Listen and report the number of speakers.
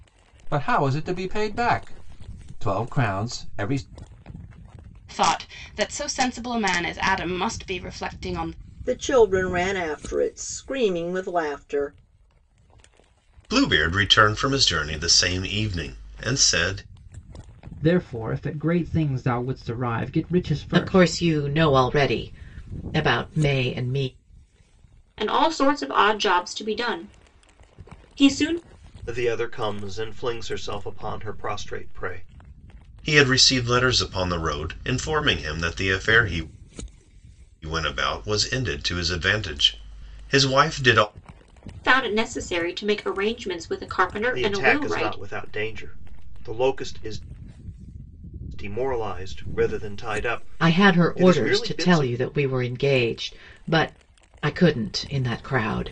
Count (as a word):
eight